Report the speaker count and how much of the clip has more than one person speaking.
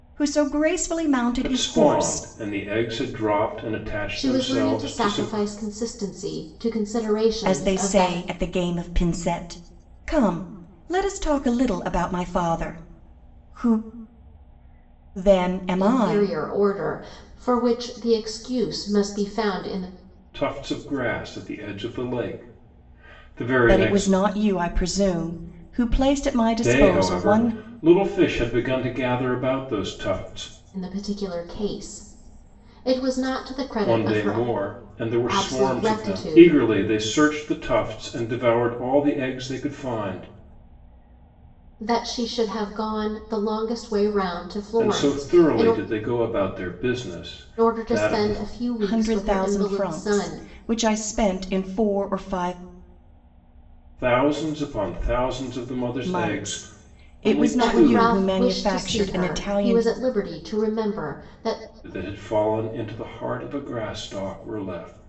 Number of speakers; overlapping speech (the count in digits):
3, about 22%